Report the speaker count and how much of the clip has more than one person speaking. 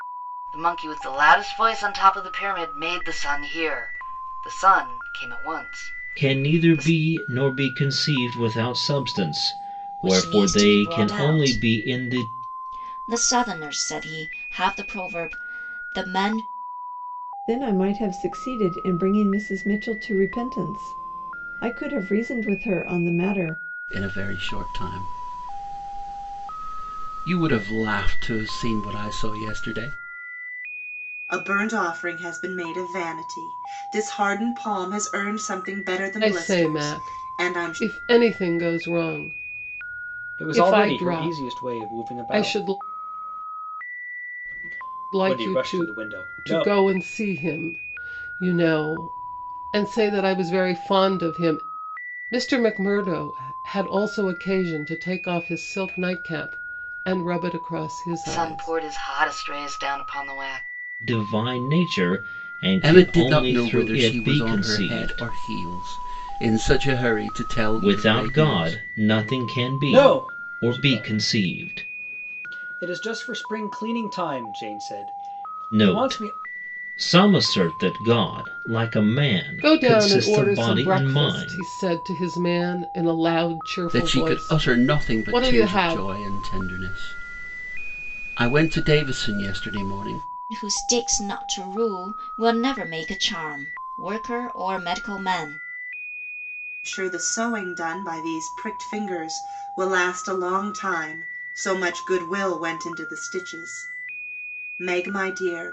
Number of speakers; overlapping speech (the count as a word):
eight, about 19%